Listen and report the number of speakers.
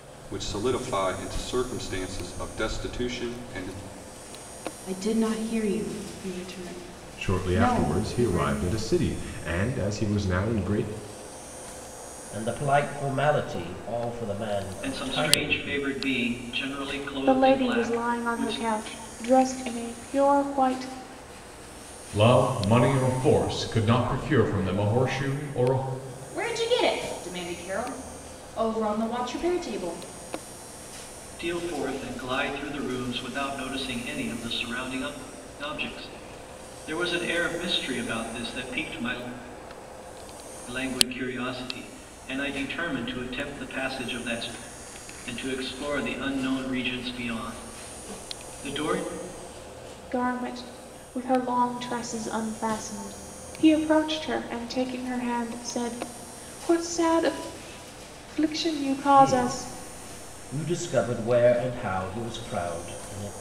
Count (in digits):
8